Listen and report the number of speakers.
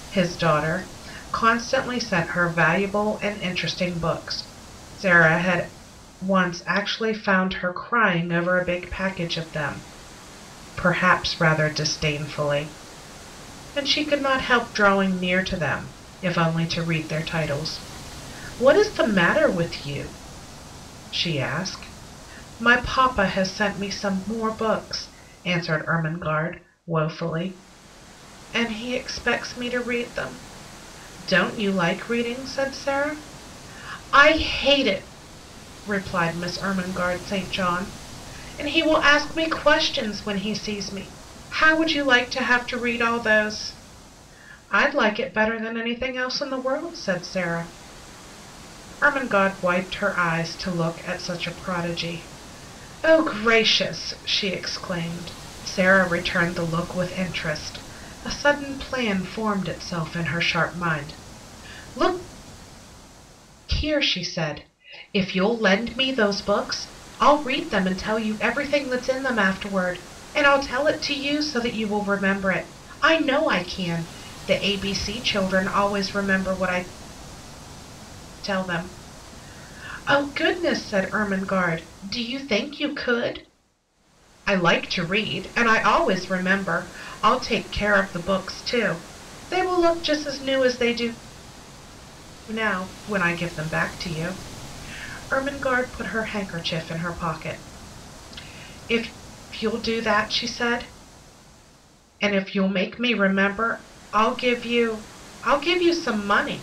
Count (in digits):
1